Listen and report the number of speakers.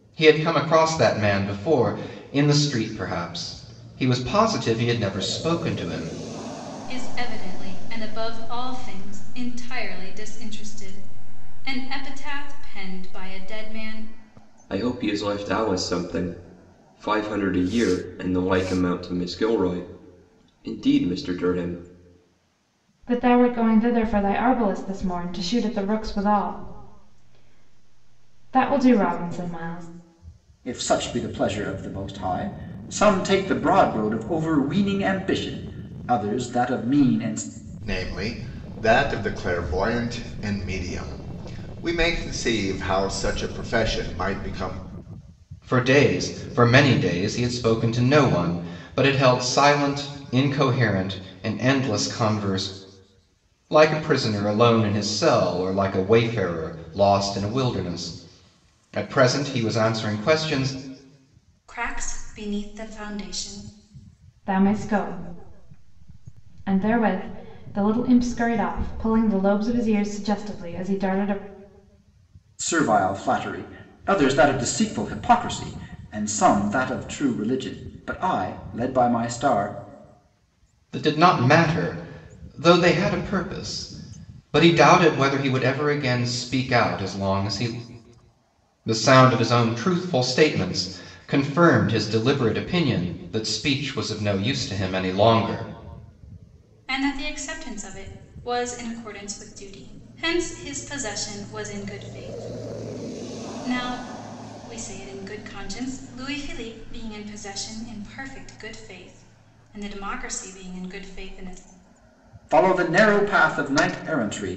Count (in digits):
6